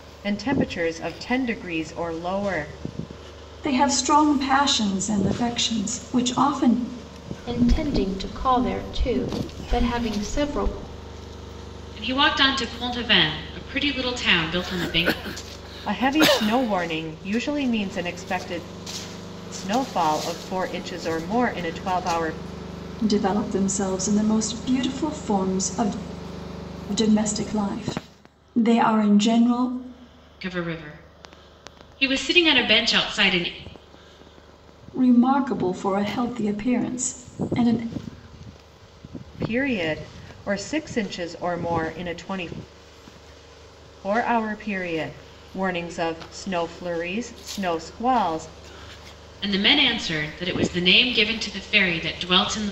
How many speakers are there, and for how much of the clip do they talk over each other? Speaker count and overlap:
four, no overlap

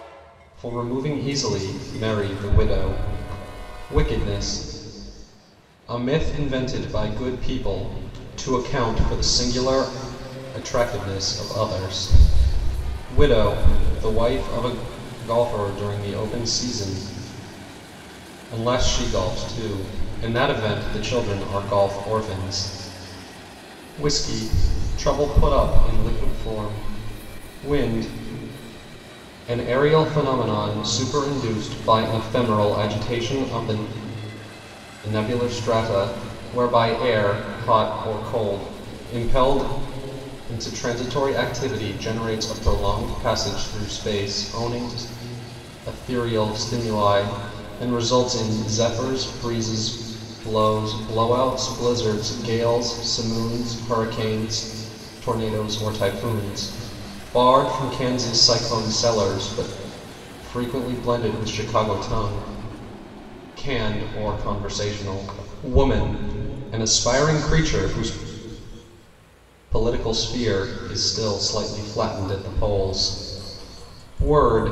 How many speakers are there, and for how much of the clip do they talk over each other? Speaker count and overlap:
one, no overlap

